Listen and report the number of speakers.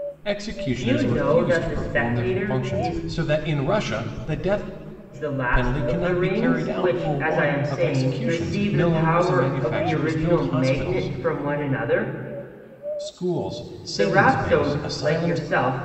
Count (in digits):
2